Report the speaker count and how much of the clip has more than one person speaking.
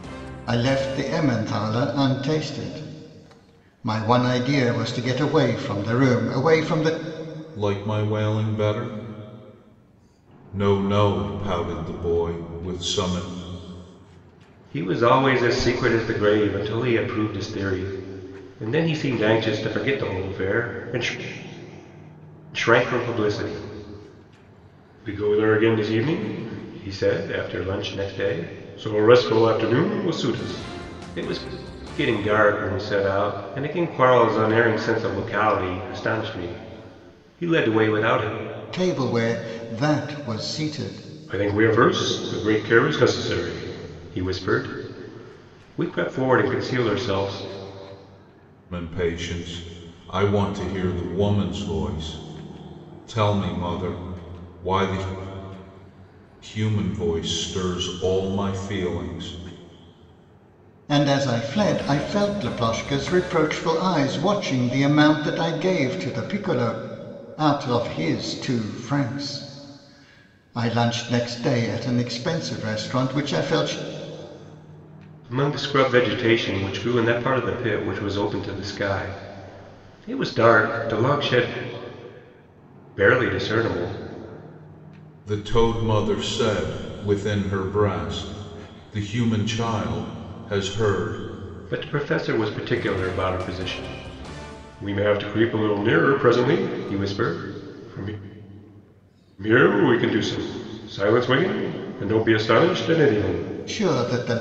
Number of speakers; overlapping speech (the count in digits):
3, no overlap